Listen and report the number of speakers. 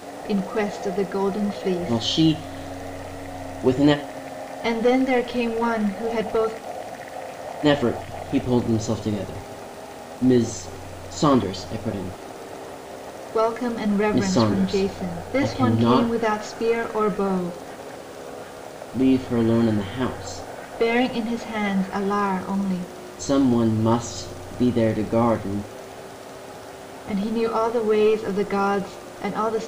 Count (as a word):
two